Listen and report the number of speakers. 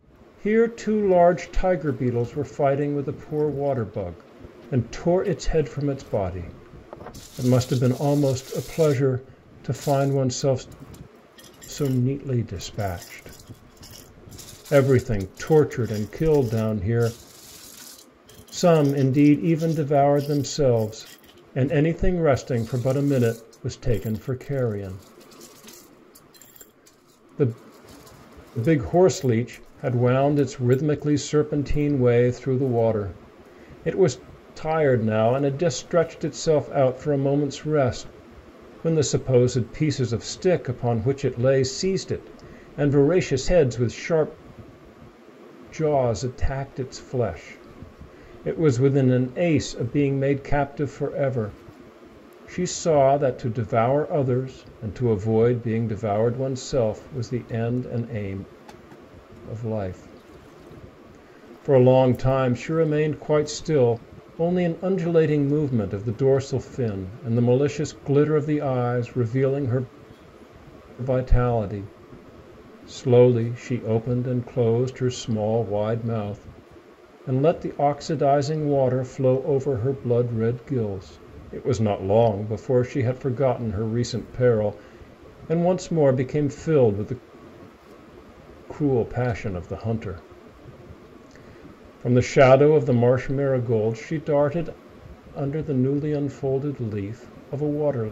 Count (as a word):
one